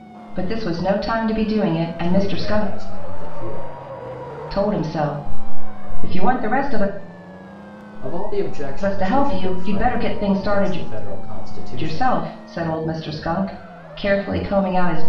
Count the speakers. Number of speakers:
two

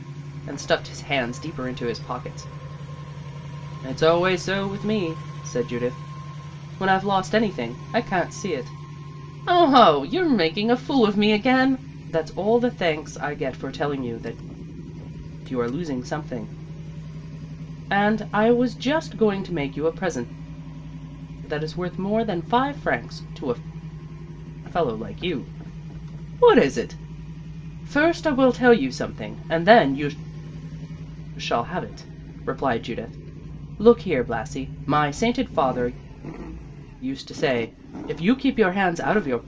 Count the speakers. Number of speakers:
one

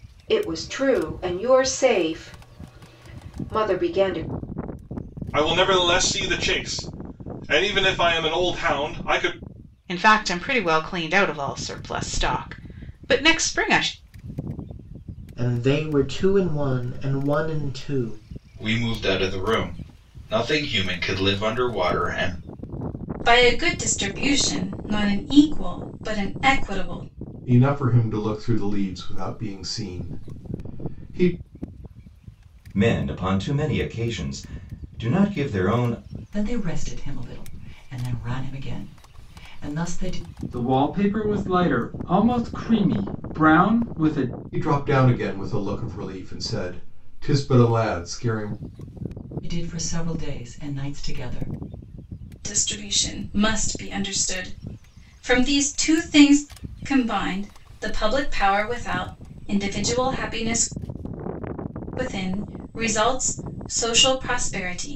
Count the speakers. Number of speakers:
ten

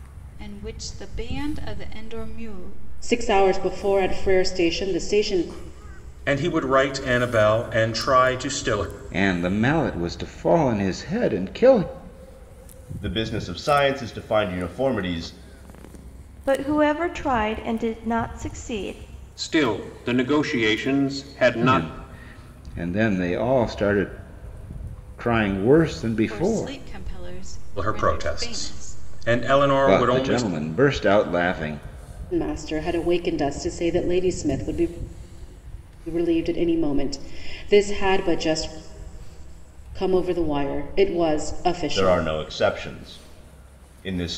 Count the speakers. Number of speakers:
seven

